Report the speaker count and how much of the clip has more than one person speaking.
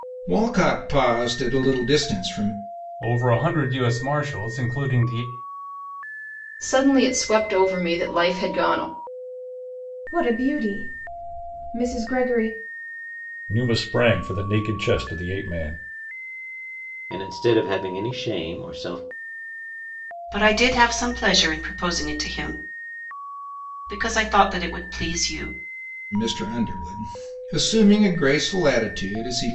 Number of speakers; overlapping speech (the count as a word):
seven, no overlap